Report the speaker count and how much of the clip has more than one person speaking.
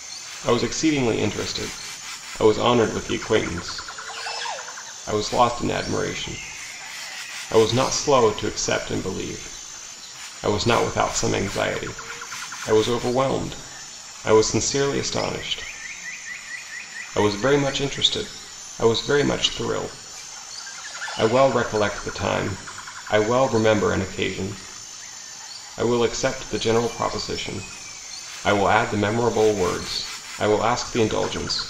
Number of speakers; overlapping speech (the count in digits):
1, no overlap